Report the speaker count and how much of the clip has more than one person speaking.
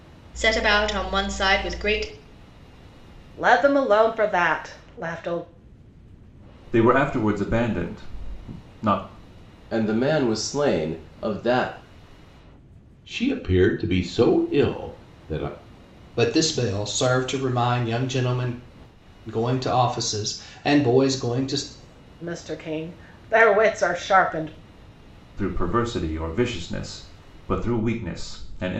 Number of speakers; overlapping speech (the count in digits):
6, no overlap